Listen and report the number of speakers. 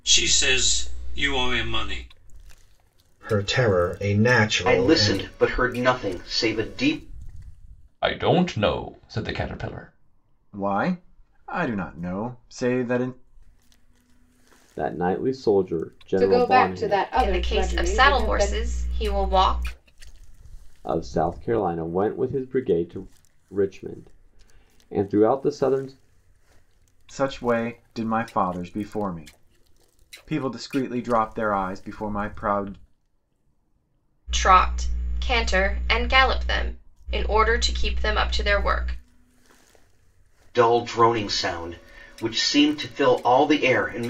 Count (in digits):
8